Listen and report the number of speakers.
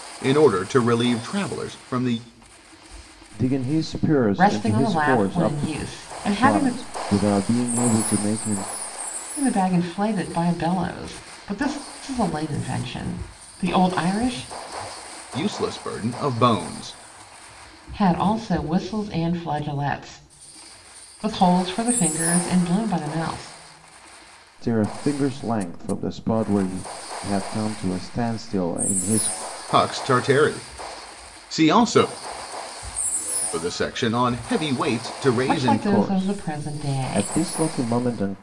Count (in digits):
3